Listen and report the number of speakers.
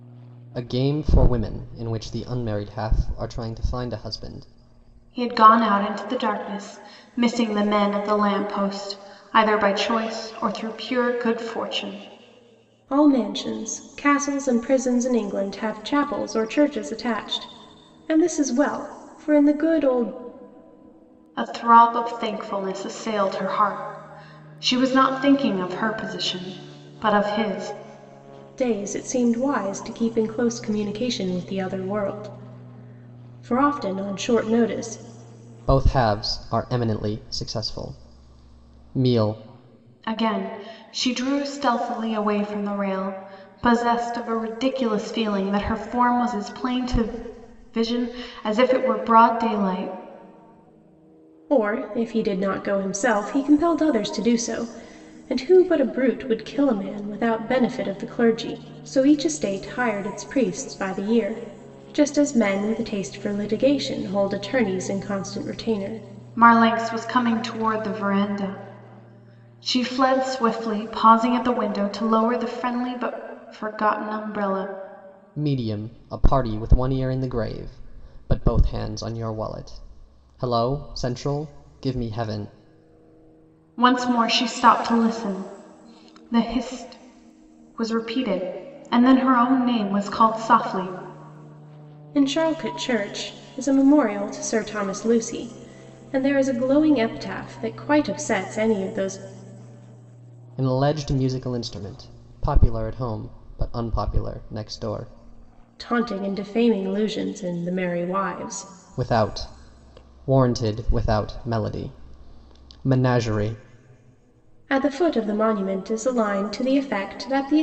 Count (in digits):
3